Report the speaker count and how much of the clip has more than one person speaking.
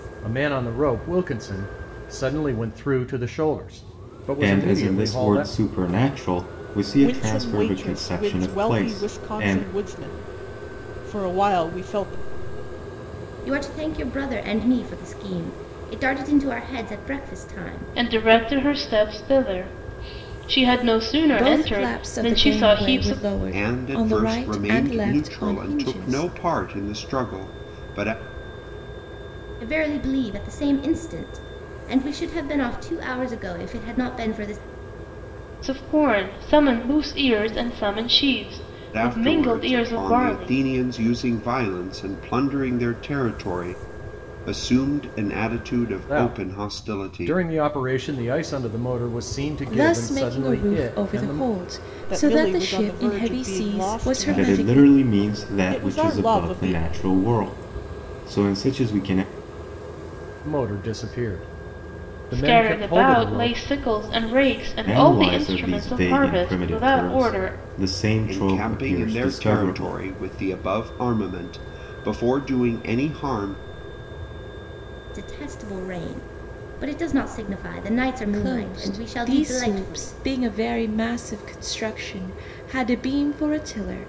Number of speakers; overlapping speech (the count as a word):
seven, about 31%